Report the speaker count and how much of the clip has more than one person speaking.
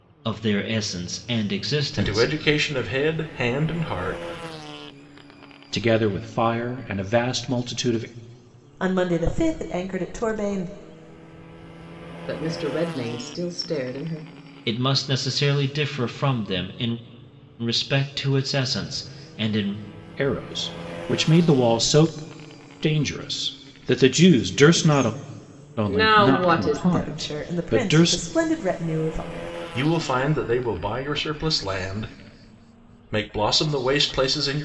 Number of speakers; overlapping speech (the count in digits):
5, about 10%